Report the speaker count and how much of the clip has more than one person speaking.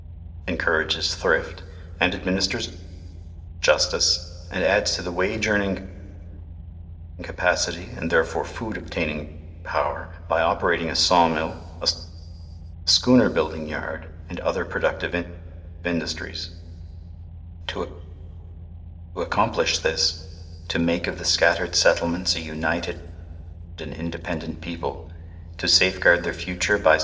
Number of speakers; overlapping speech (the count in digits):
1, no overlap